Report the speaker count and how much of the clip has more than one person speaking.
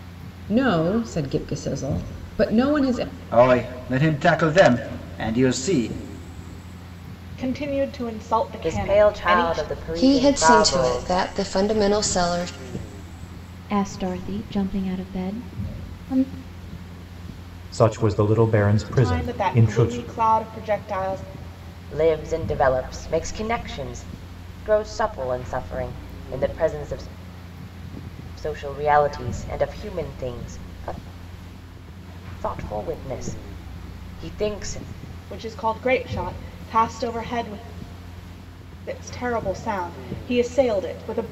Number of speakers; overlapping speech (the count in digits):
7, about 9%